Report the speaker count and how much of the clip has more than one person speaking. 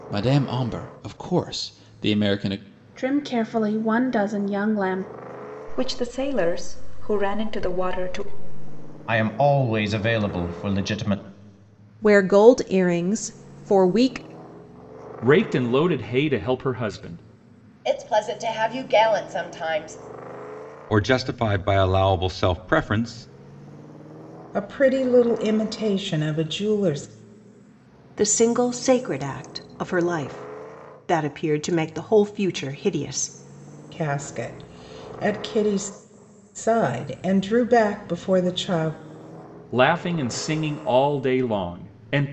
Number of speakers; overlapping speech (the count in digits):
10, no overlap